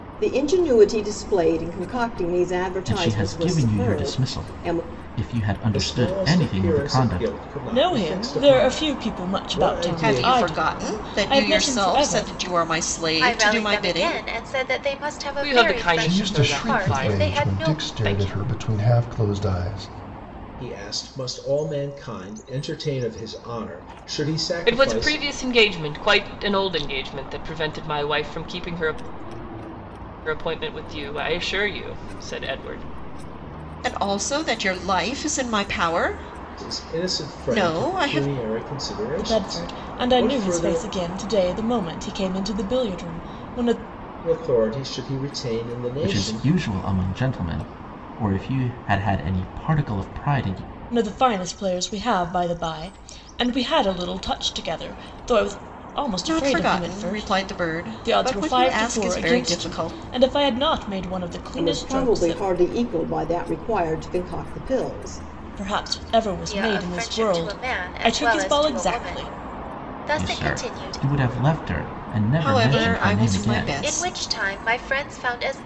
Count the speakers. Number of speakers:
8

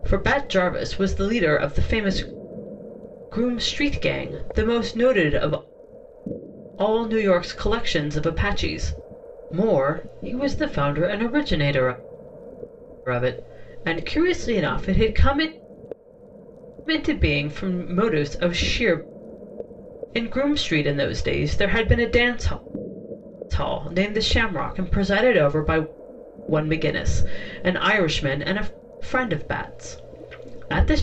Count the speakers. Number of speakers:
1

